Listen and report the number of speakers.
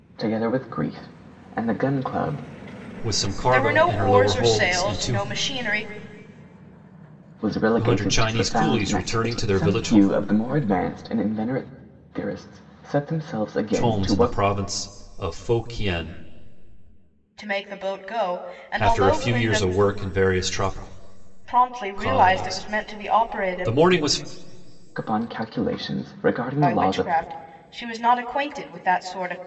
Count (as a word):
three